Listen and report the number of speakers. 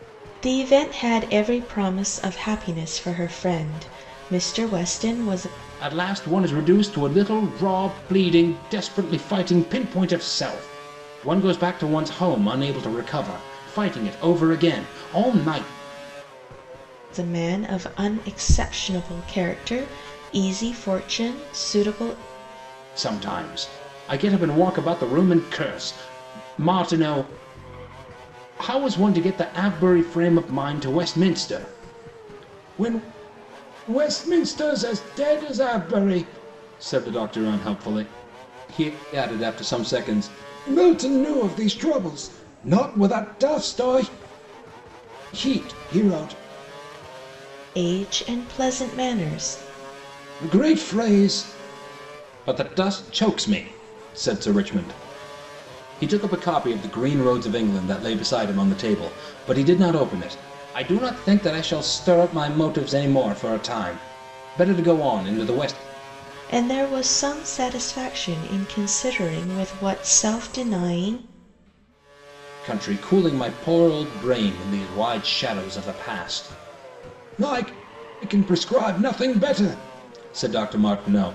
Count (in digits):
2